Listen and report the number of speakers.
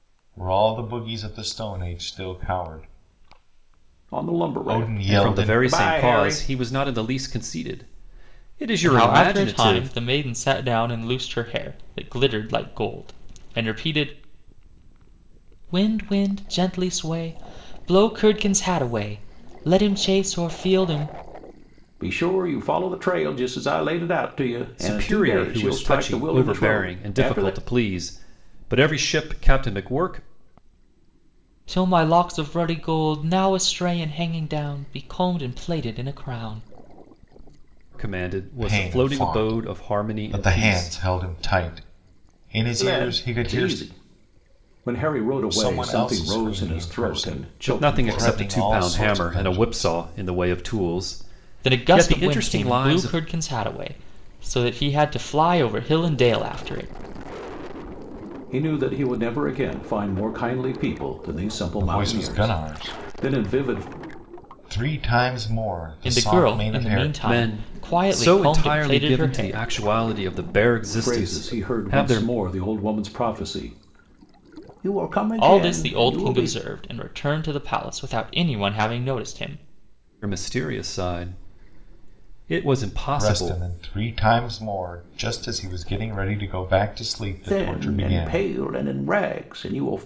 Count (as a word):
four